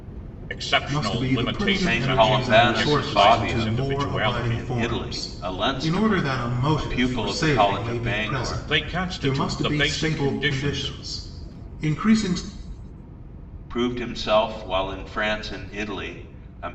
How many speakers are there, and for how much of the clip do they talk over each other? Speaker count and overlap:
3, about 55%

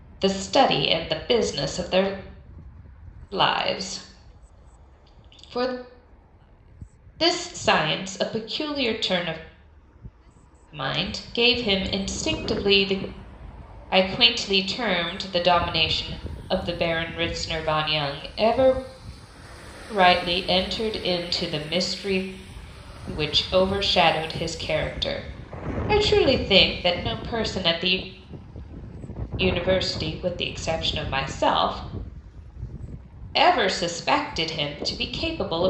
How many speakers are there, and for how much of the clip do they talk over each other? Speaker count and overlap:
1, no overlap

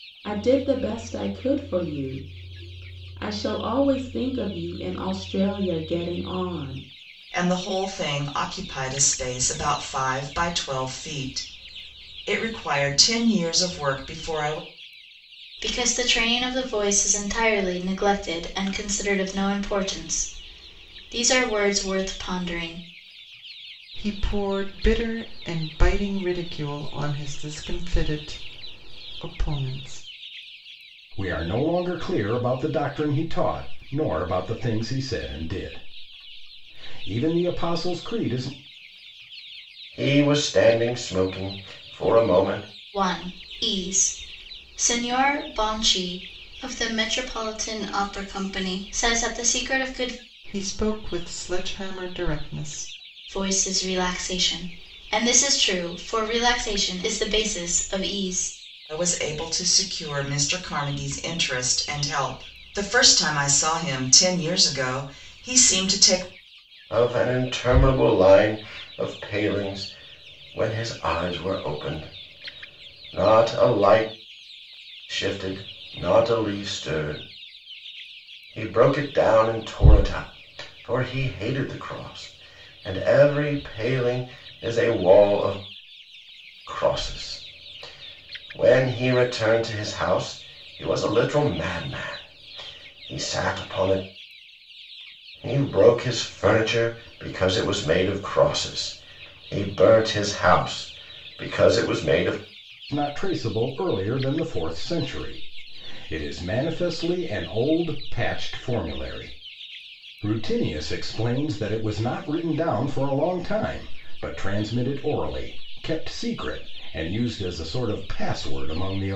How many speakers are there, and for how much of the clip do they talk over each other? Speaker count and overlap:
6, no overlap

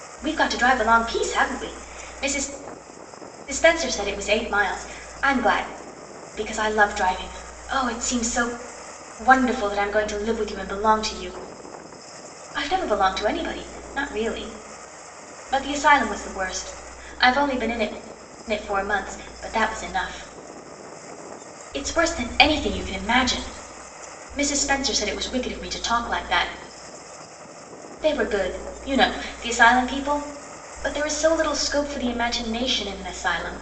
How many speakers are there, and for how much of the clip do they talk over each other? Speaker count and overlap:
1, no overlap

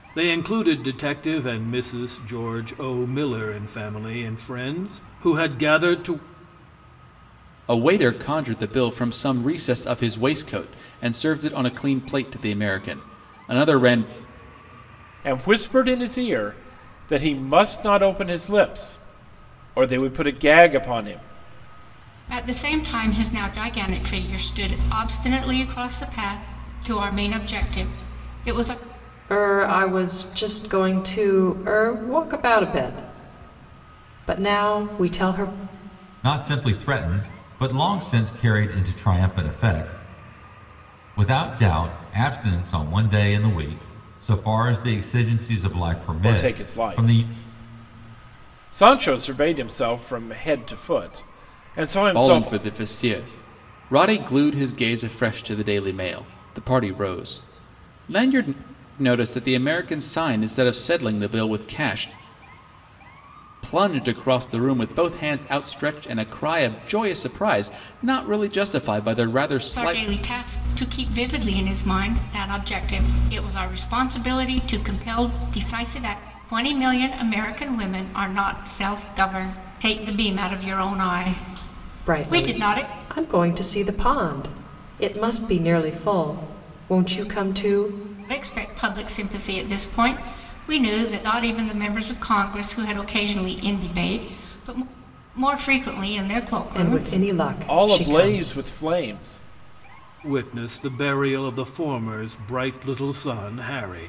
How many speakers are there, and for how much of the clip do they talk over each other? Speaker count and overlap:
6, about 4%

